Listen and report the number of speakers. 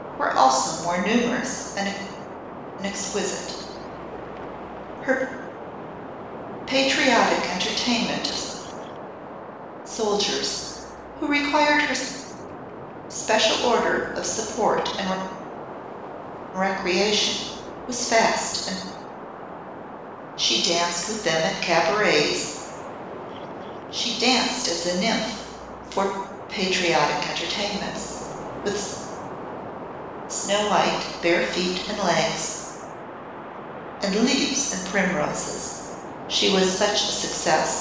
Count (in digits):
1